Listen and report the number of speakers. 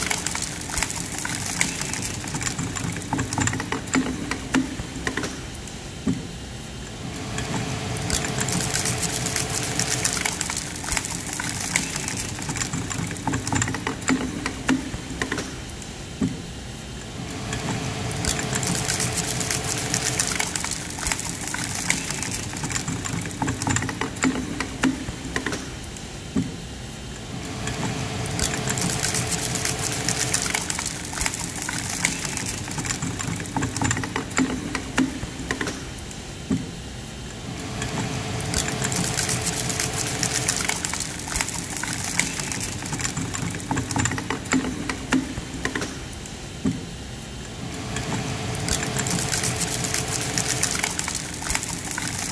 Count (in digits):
0